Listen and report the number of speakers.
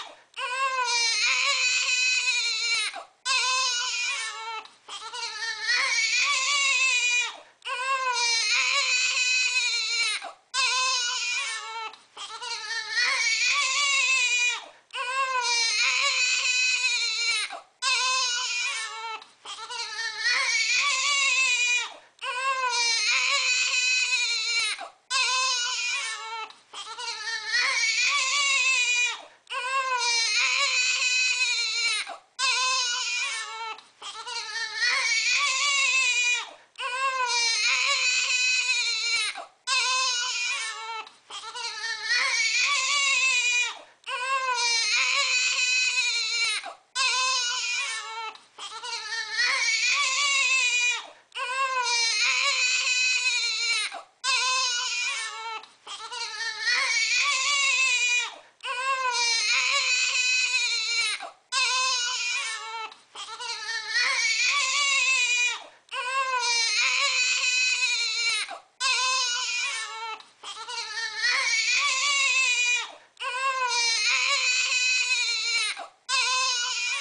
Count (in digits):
0